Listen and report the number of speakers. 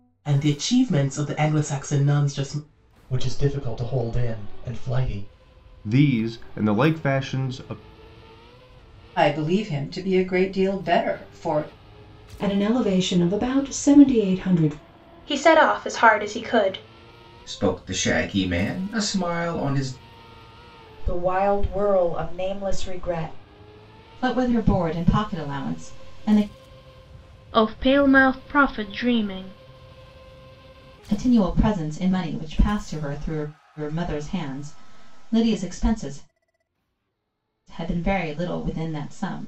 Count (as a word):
ten